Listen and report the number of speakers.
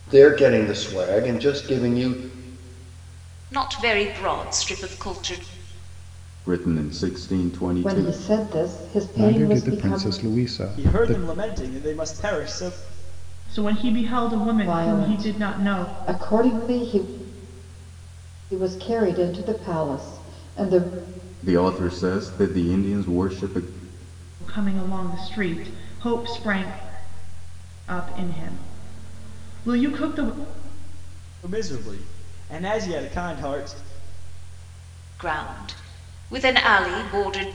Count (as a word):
seven